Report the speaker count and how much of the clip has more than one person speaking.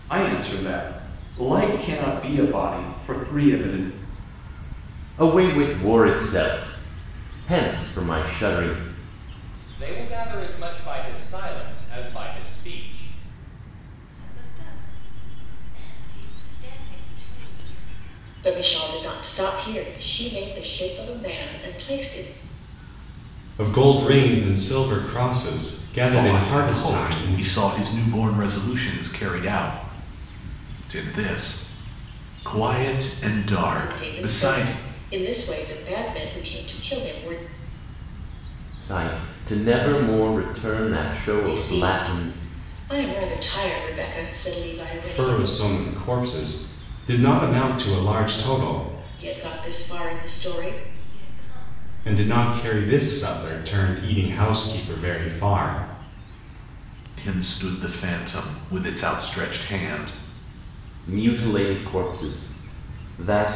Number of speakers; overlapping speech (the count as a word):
seven, about 9%